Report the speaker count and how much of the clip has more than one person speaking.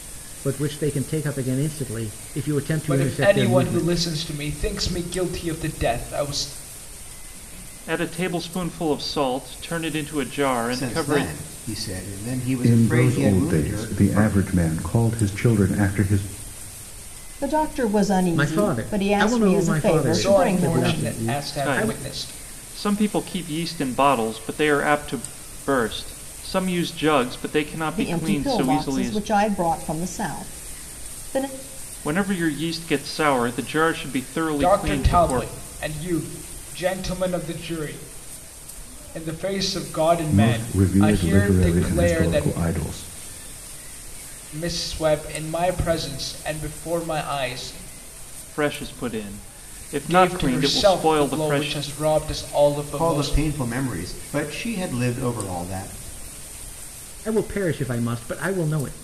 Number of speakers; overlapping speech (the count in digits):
6, about 25%